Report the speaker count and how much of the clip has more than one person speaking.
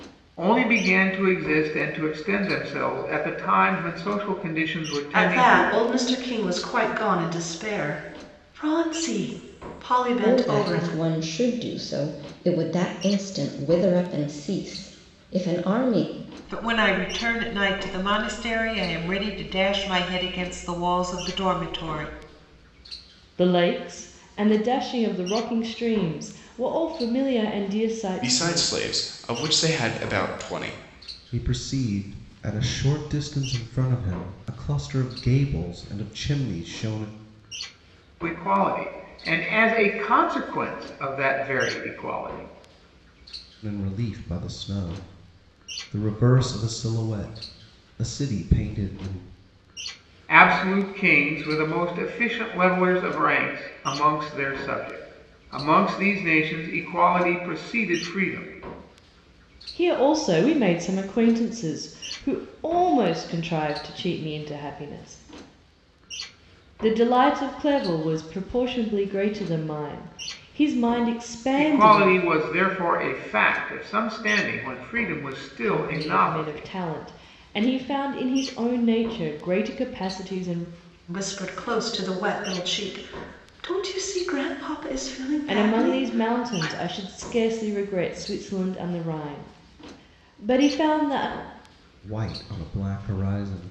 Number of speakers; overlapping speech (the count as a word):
seven, about 5%